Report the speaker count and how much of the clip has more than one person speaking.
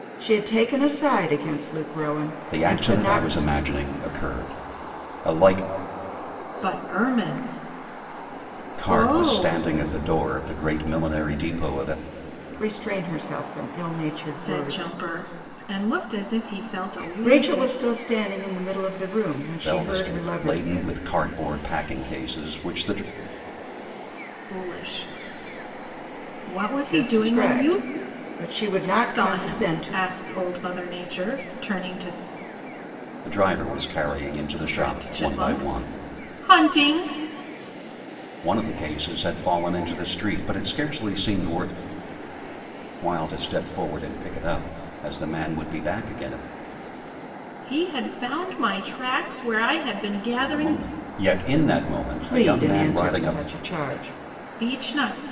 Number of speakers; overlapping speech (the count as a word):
three, about 16%